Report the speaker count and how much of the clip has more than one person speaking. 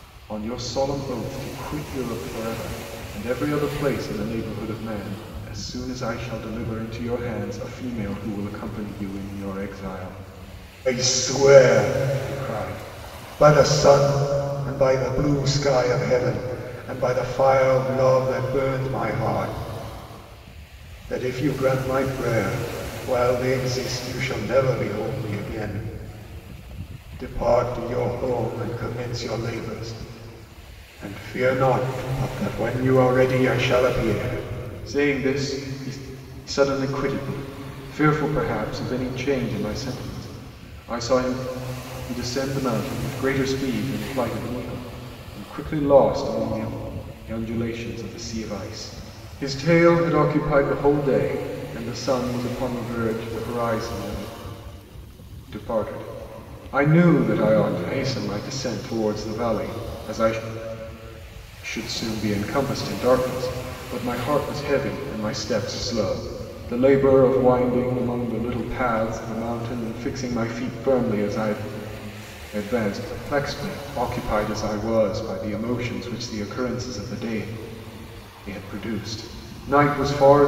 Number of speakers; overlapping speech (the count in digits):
1, no overlap